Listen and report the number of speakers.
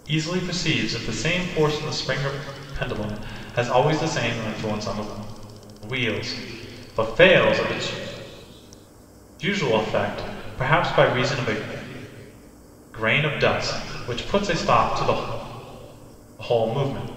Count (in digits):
1